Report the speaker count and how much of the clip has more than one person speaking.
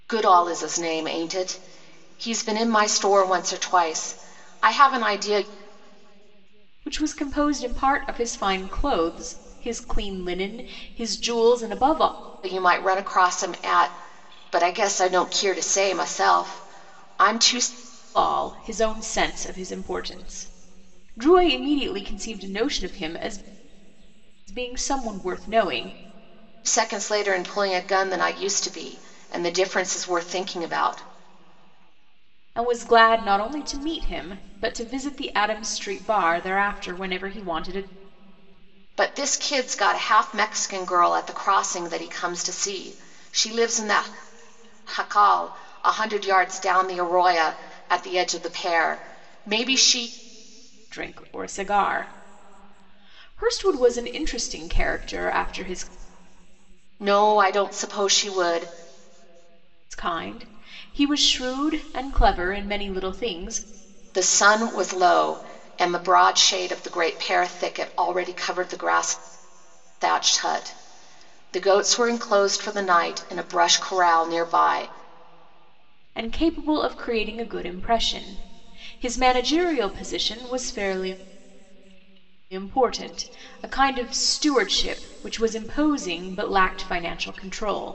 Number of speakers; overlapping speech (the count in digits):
2, no overlap